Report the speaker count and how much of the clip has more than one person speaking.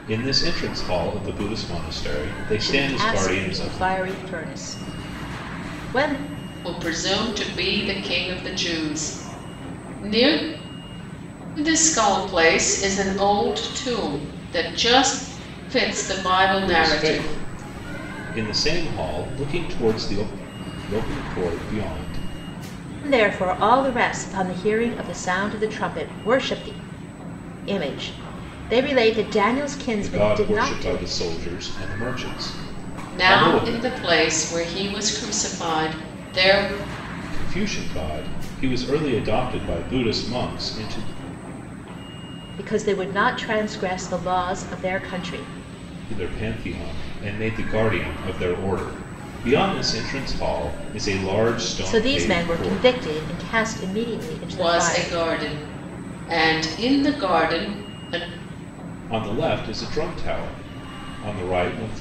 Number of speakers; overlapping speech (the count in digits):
3, about 10%